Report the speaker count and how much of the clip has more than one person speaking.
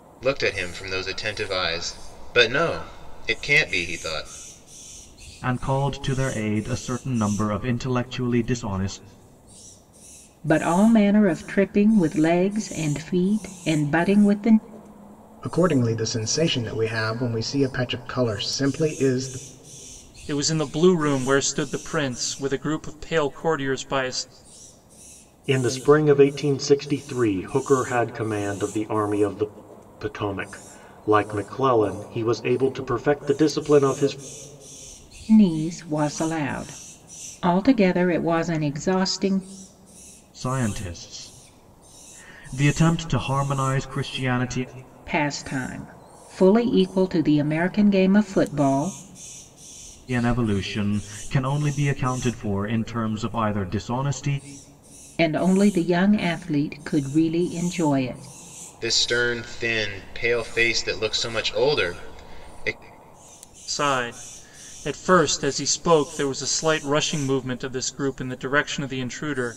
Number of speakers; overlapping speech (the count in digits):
6, no overlap